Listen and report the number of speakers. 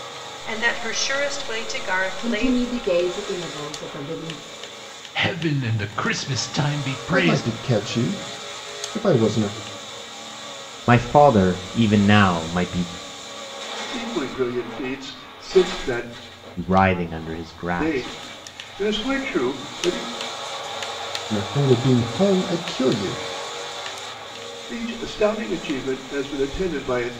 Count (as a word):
six